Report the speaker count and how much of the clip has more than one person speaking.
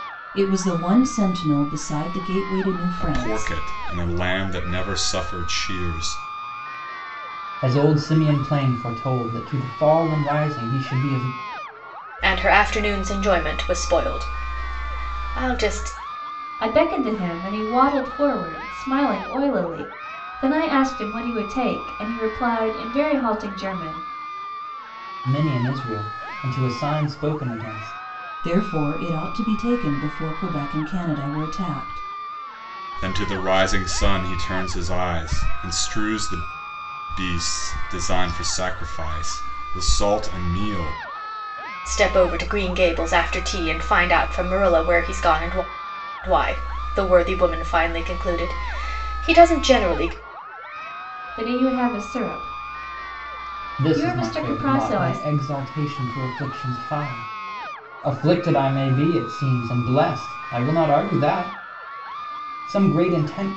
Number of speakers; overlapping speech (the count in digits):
5, about 3%